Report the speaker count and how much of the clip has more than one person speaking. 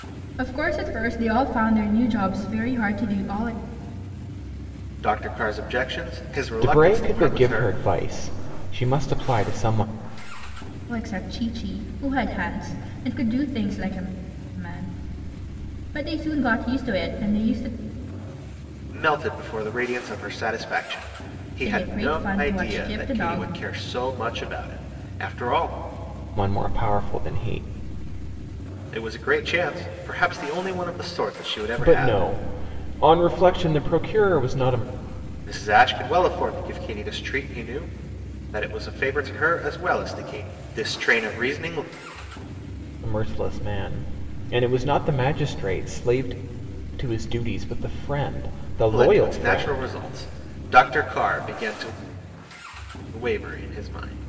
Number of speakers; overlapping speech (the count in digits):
3, about 8%